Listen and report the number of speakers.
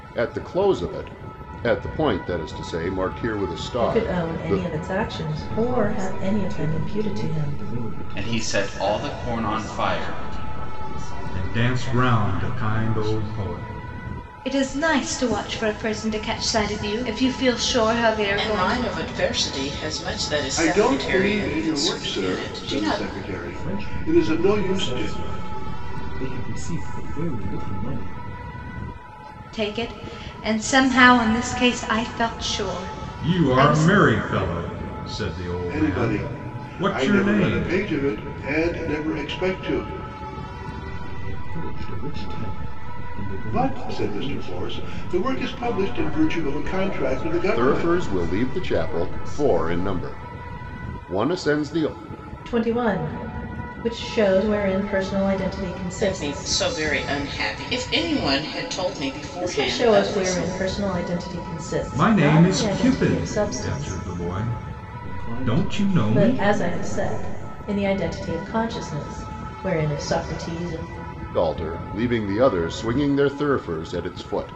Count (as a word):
nine